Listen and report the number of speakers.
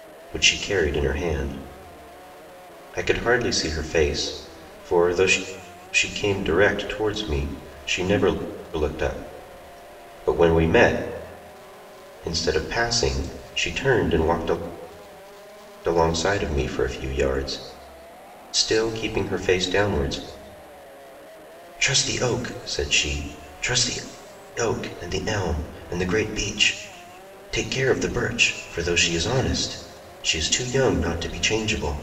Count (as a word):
one